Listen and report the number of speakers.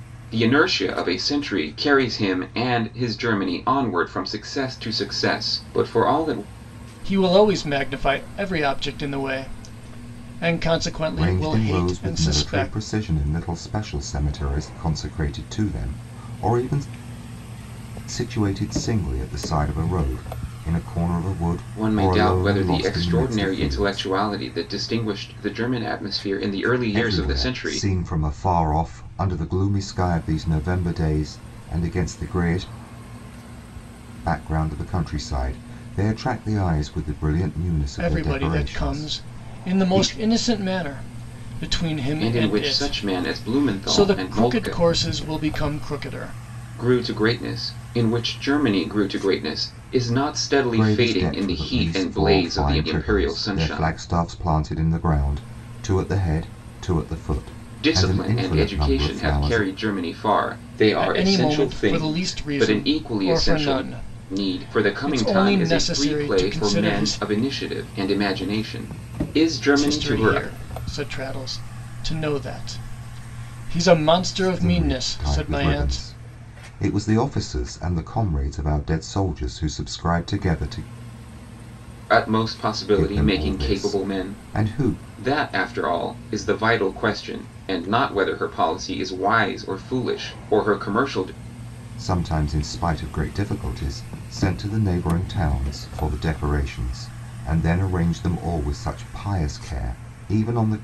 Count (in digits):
3